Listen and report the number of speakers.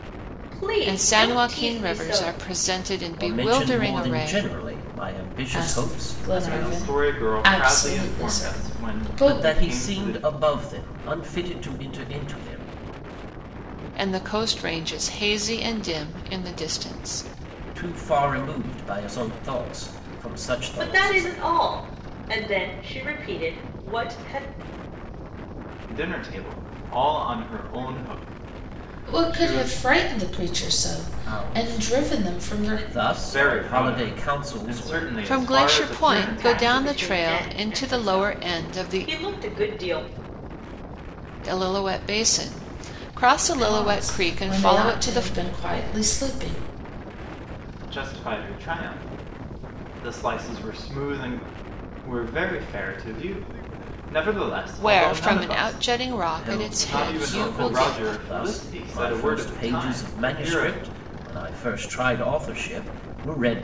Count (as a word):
five